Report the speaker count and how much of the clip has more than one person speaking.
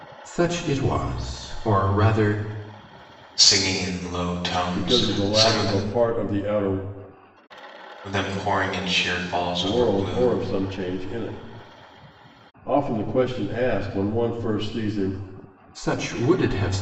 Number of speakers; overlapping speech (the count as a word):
three, about 10%